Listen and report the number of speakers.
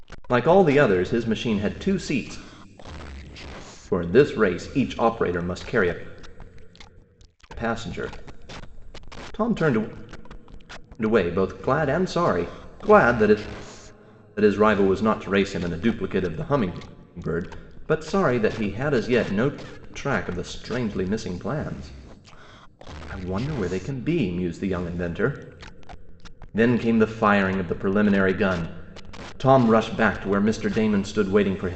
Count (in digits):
1